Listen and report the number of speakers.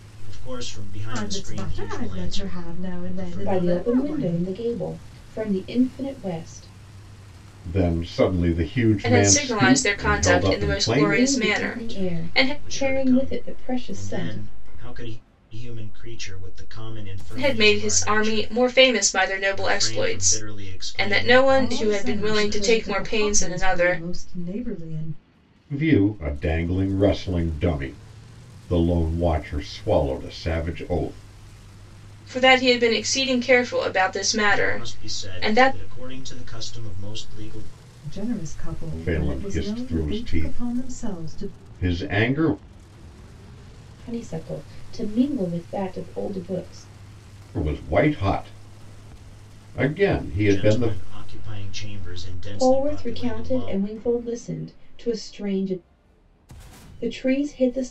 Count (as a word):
five